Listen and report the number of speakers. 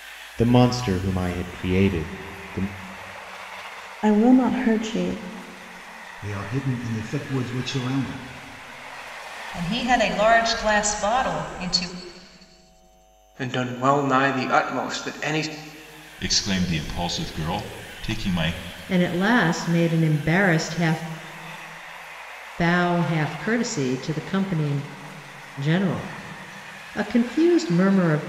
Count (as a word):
seven